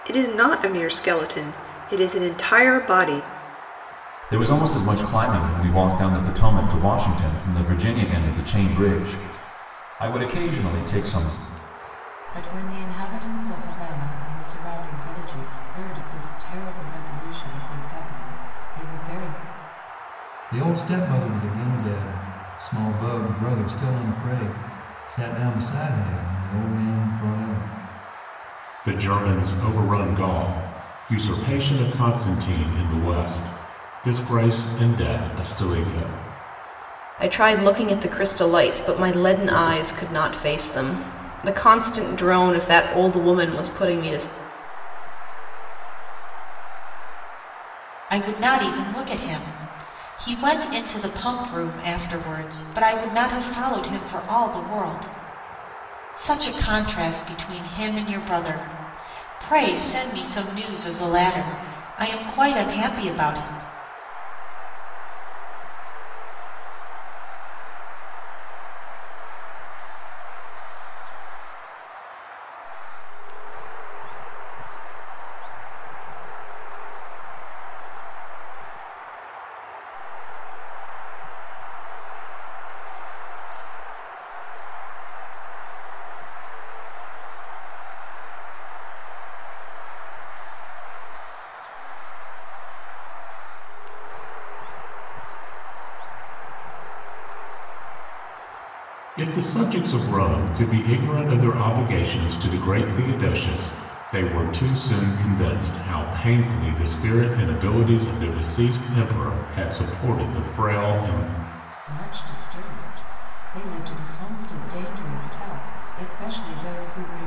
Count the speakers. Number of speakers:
eight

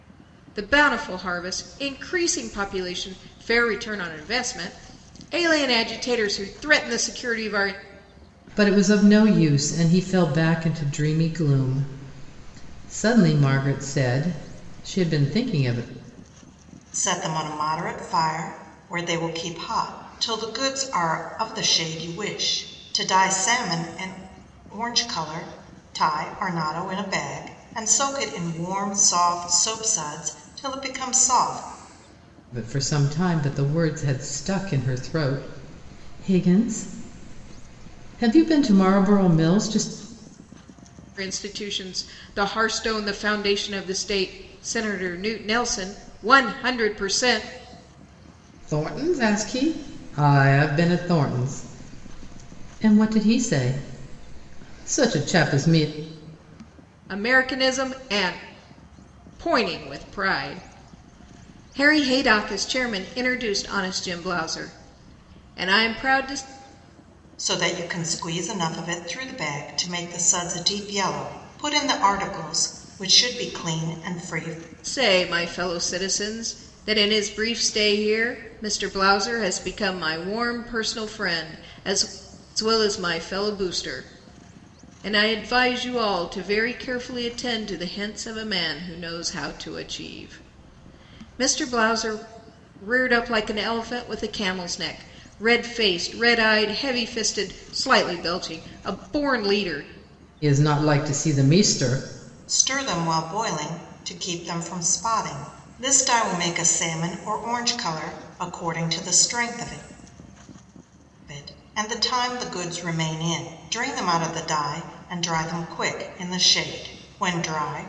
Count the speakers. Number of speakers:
three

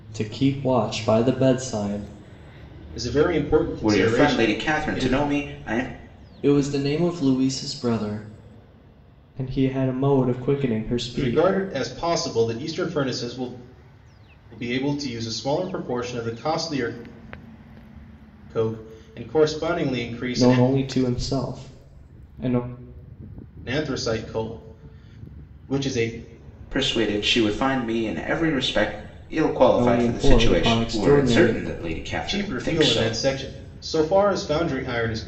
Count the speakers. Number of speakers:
three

